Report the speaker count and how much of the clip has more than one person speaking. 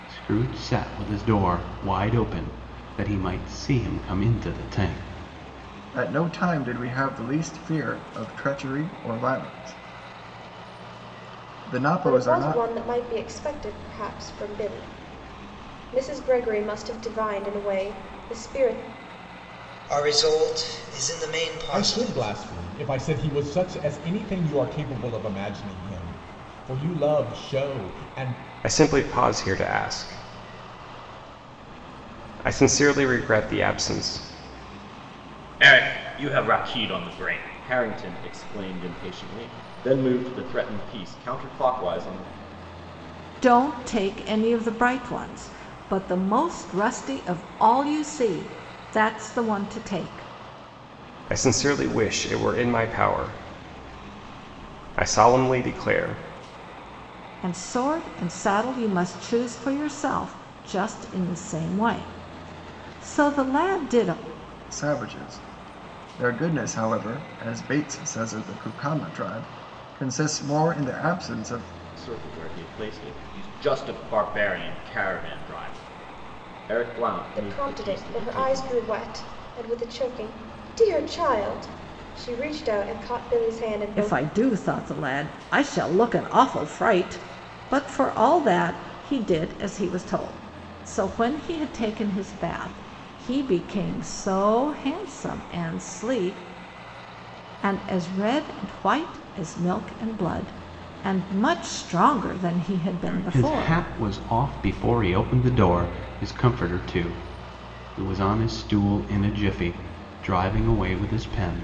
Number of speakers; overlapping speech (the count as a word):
eight, about 4%